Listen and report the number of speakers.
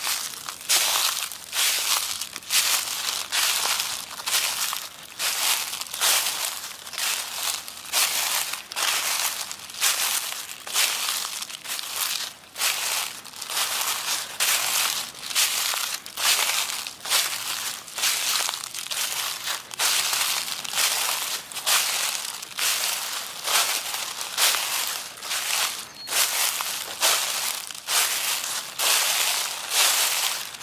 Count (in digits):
0